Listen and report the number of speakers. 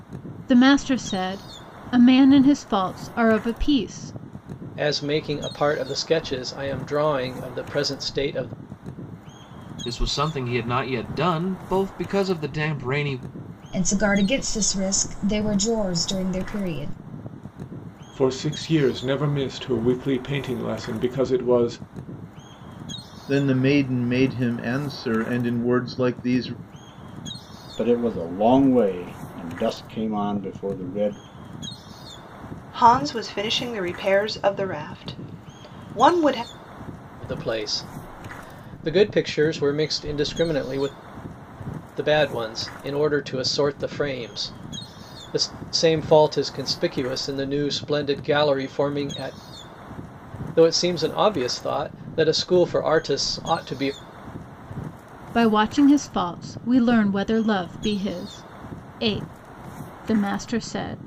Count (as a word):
eight